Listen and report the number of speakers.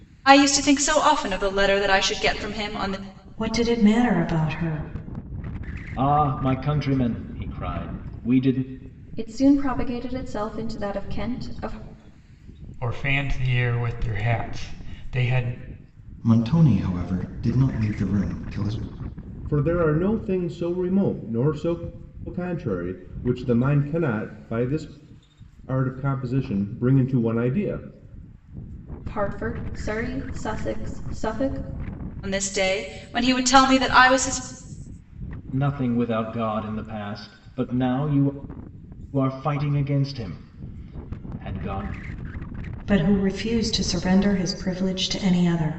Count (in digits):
7